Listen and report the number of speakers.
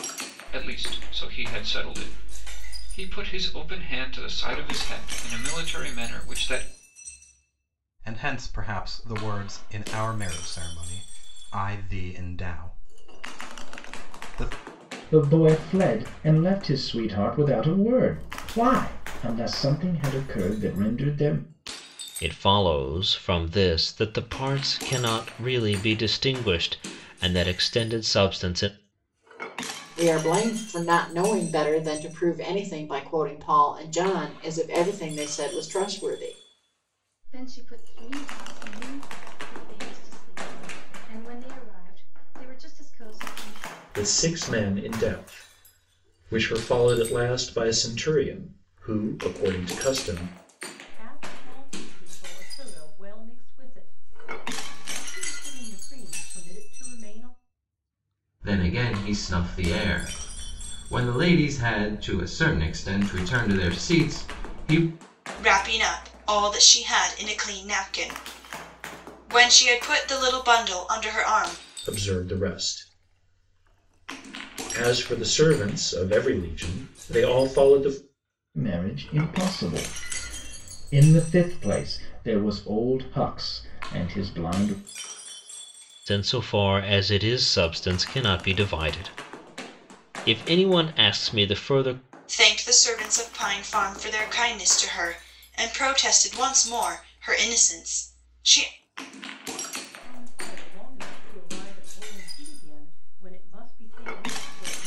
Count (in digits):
10